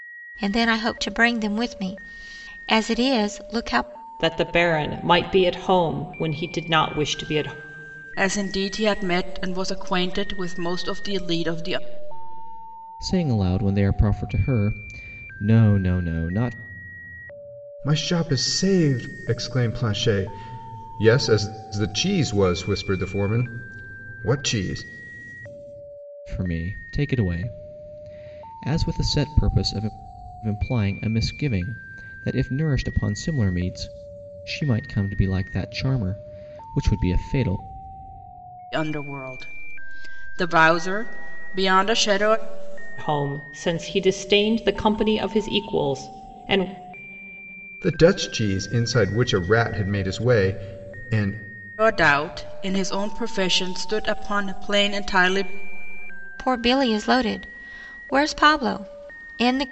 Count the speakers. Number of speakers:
five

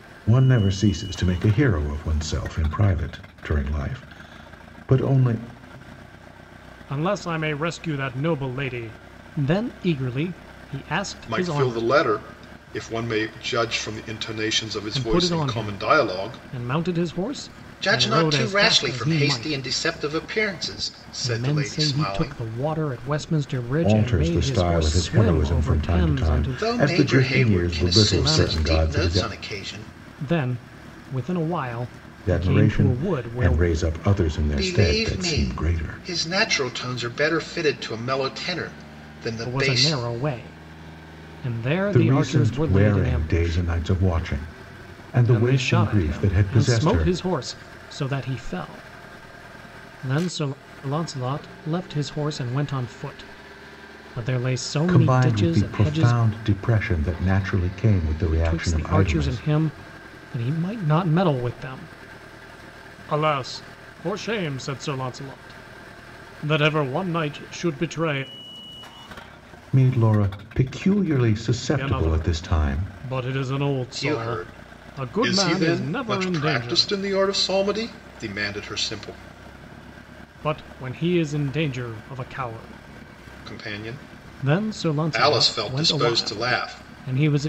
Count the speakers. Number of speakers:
three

